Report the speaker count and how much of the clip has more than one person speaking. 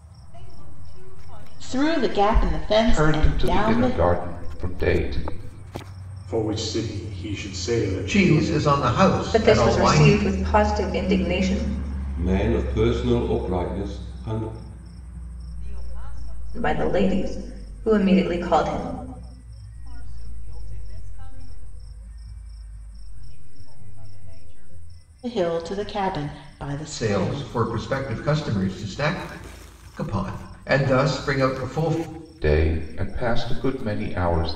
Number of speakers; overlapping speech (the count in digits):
7, about 14%